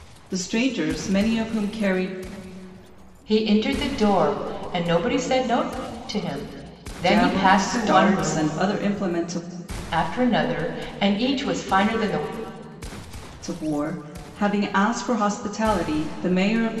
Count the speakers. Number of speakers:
2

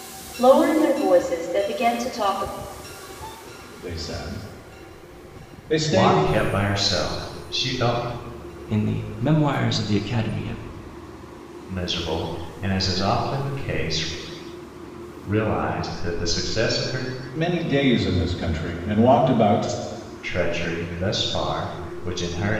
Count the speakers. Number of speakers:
4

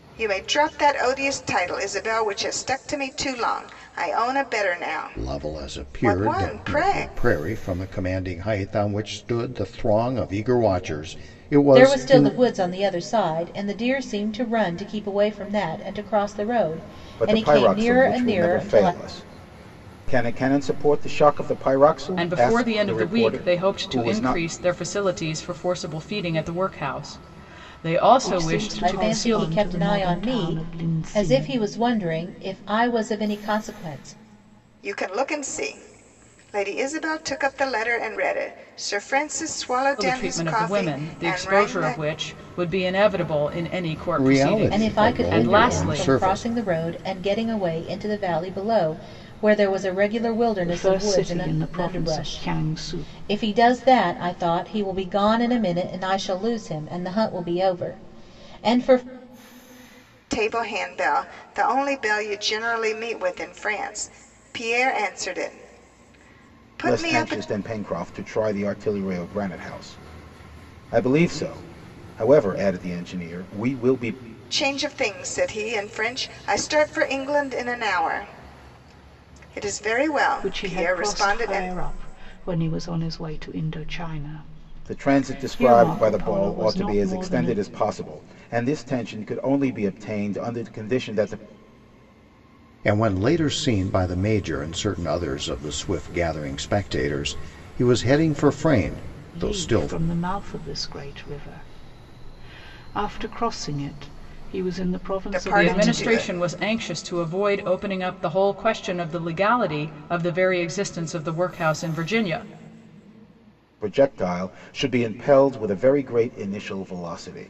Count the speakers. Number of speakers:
6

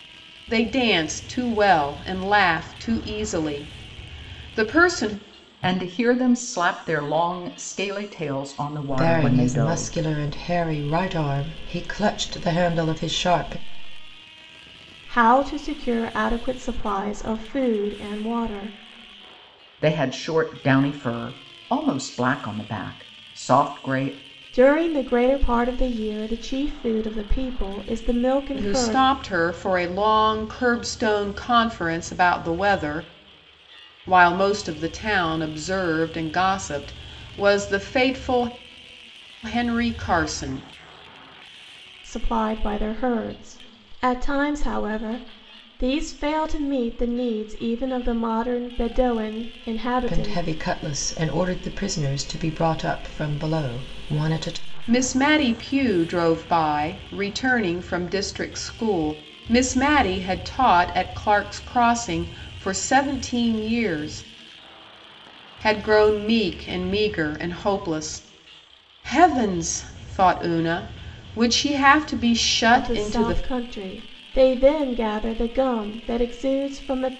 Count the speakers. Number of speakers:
4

